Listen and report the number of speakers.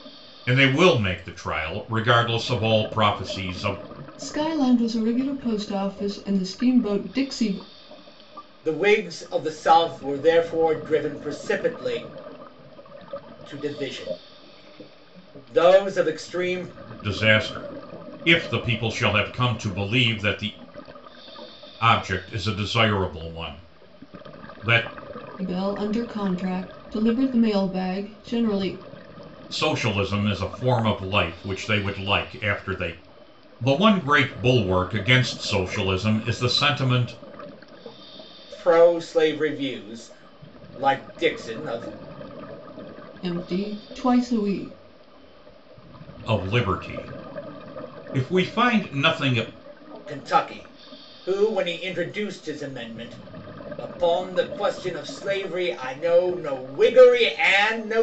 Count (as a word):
three